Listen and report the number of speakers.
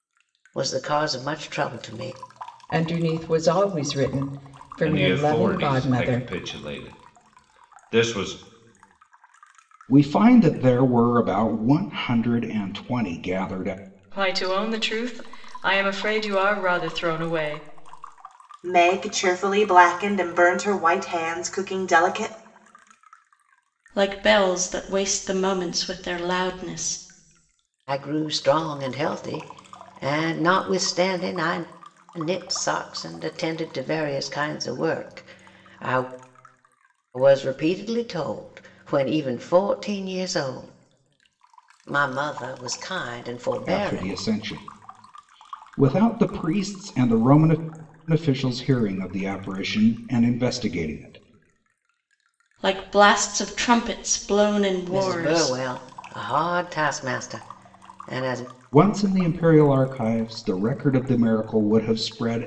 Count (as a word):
seven